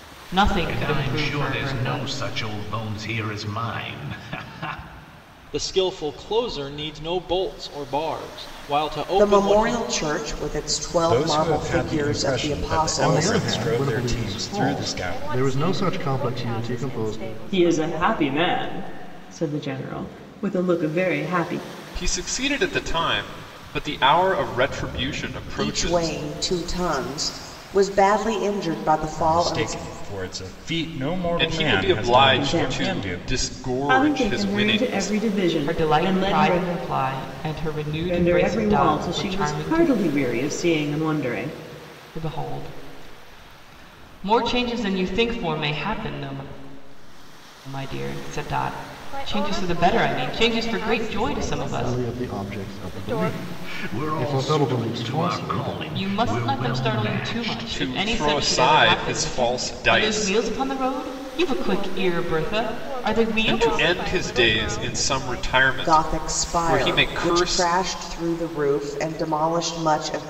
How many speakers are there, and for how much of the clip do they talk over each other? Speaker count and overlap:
9, about 49%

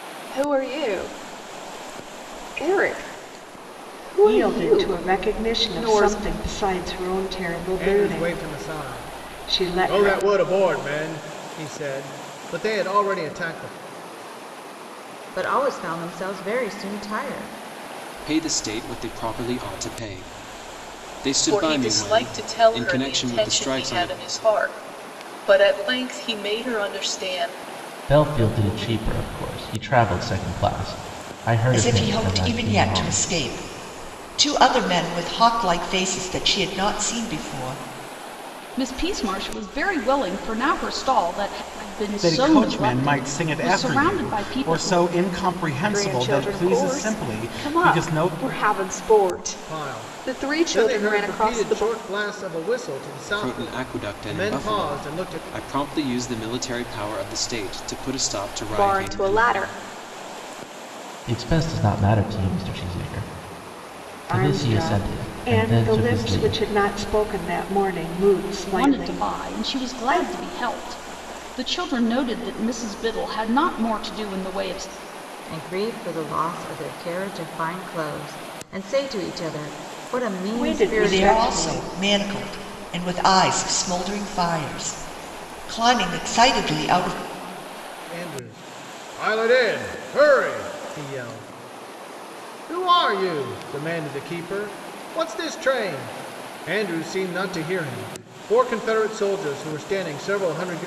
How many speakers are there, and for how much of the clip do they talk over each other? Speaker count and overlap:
10, about 25%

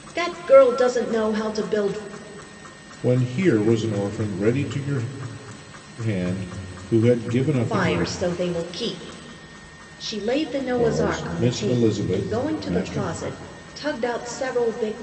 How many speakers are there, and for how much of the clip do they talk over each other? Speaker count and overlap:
2, about 20%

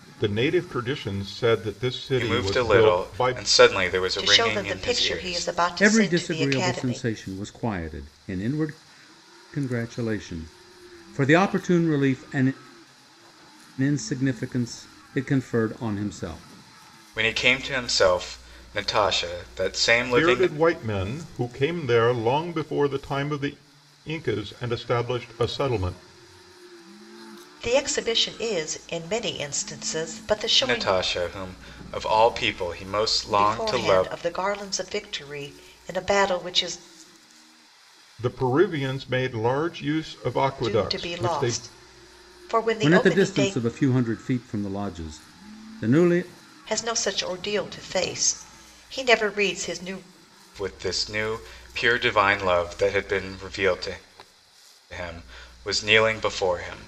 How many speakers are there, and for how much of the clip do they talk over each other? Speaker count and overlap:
4, about 13%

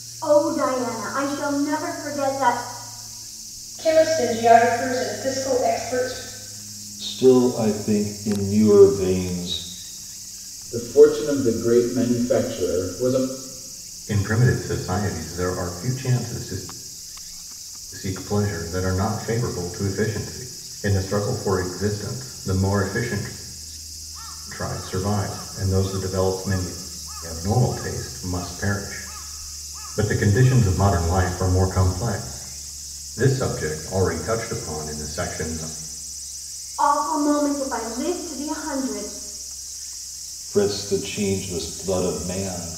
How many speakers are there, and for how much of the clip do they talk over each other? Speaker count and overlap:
5, no overlap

